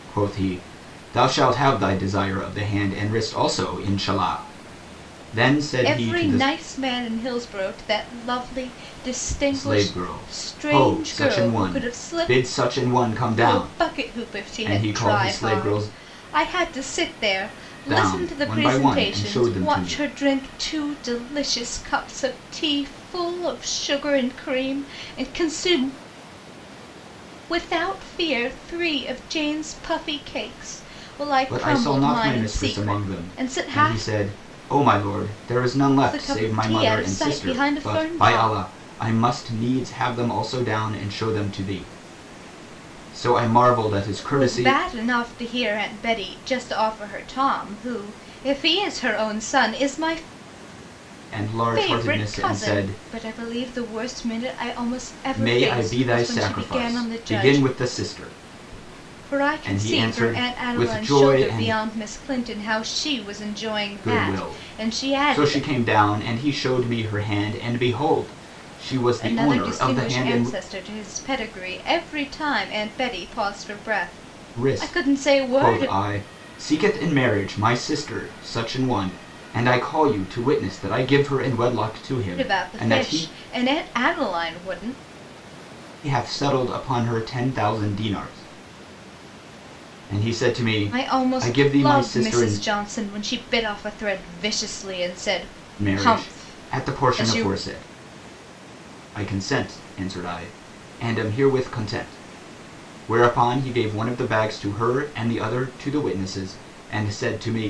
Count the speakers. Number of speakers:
2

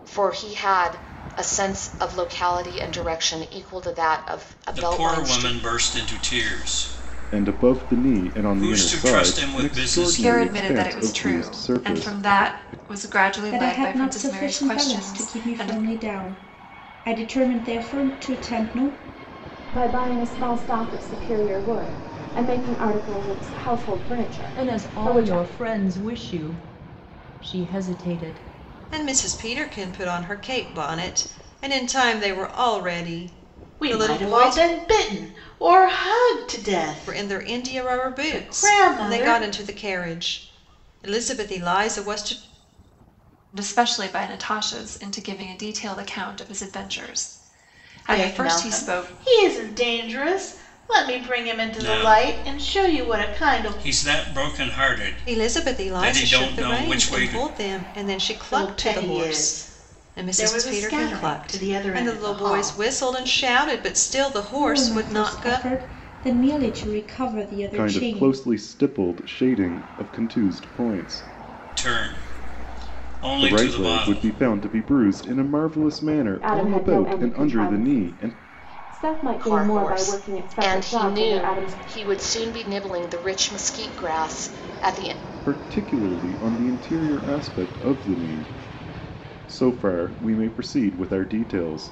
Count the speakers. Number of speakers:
9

